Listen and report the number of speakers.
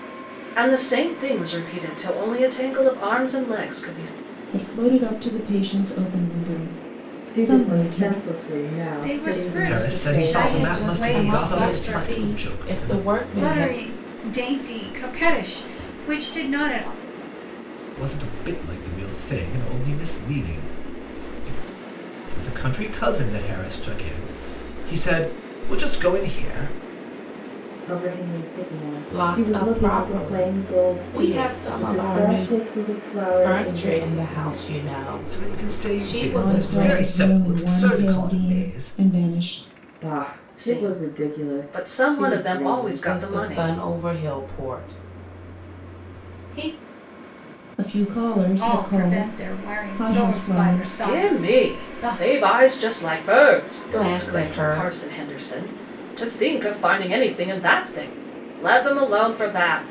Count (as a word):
six